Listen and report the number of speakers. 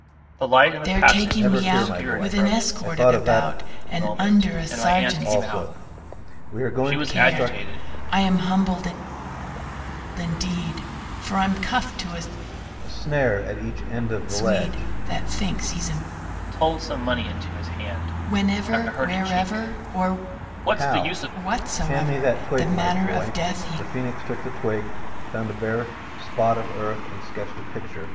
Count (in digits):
3